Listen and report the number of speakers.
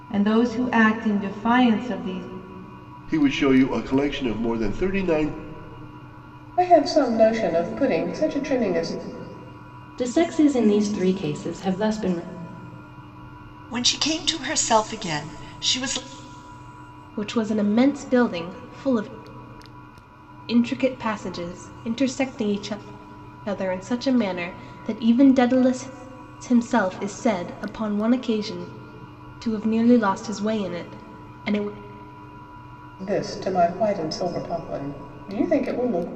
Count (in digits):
6